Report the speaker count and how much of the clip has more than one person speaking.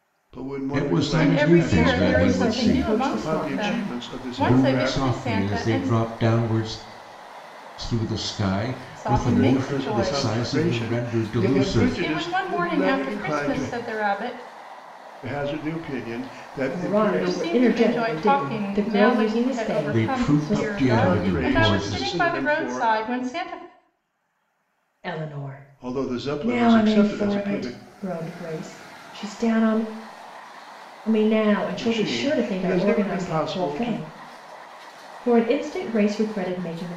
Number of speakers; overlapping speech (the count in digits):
4, about 55%